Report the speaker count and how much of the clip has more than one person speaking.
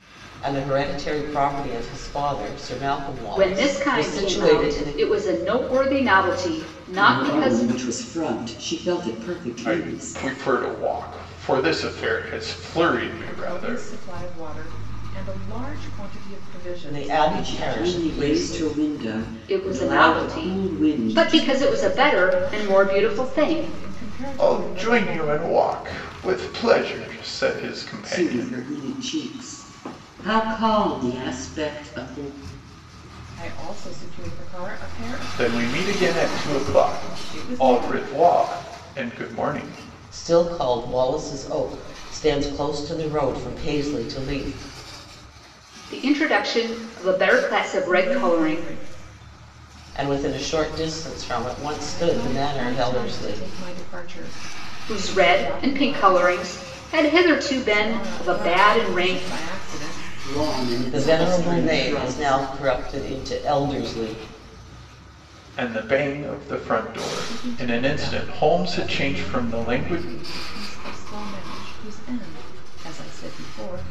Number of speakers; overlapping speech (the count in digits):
5, about 33%